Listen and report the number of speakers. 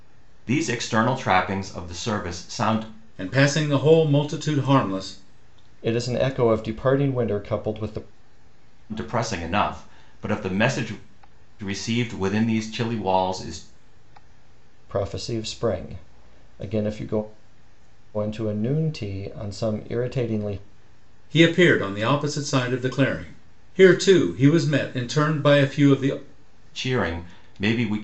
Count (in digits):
3